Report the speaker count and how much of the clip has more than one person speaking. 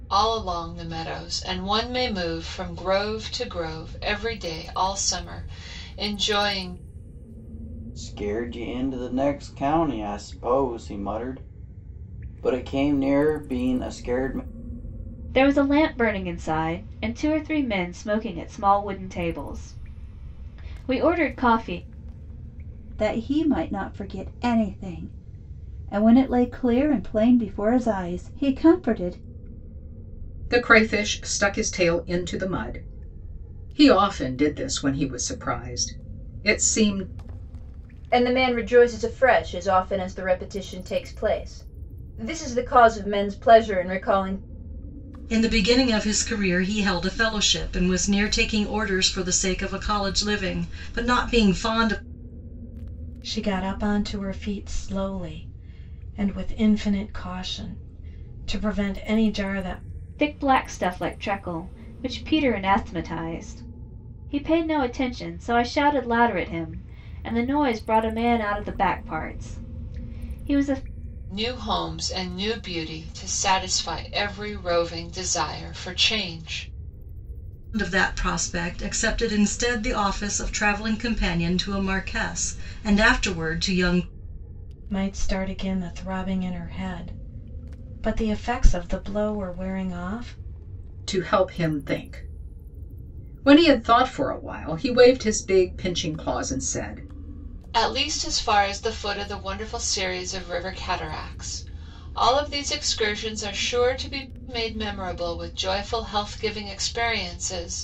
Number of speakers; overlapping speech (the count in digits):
8, no overlap